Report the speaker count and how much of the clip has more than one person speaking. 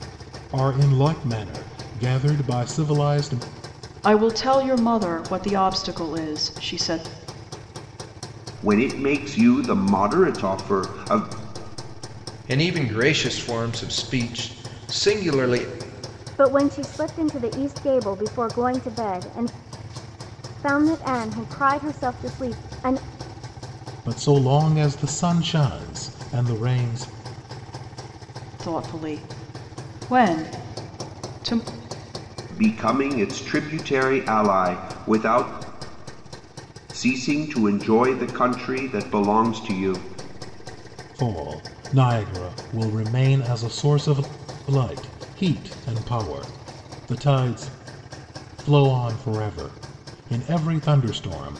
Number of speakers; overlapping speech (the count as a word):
five, no overlap